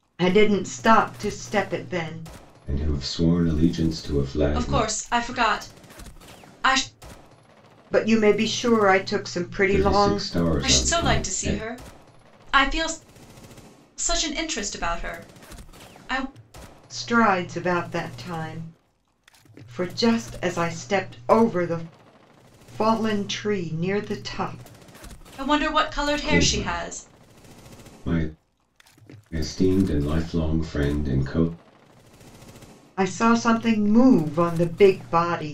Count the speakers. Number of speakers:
three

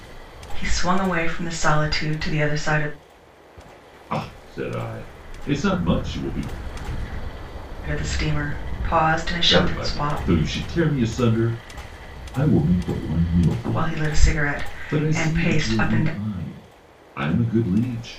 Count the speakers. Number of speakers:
two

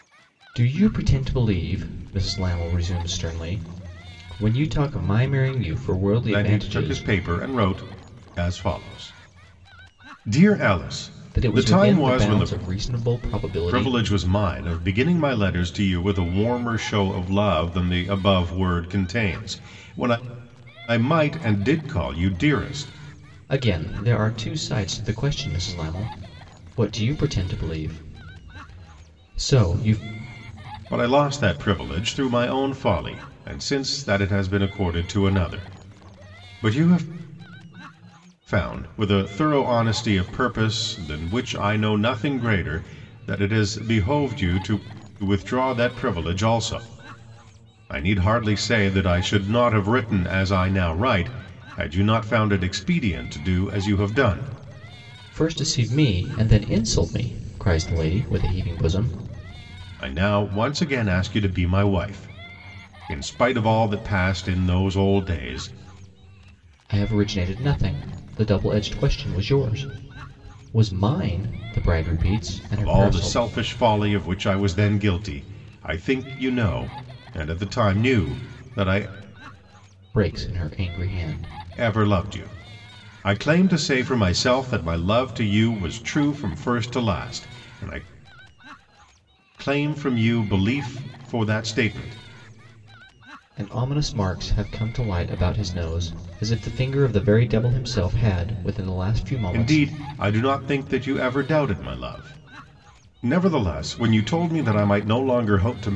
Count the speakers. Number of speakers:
two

